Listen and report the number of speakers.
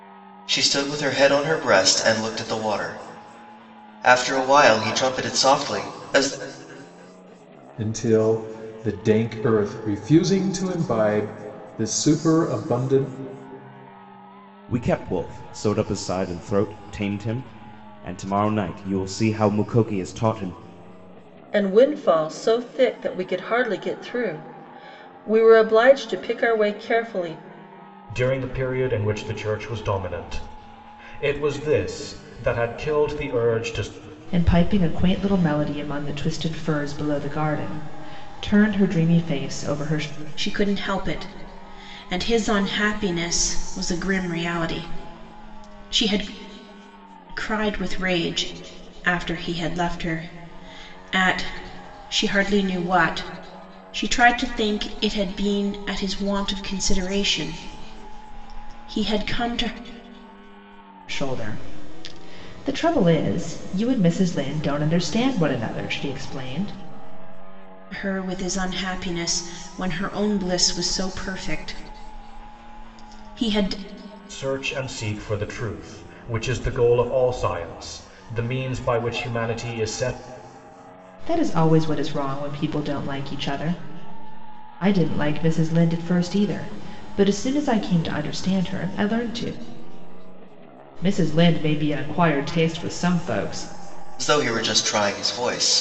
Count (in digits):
7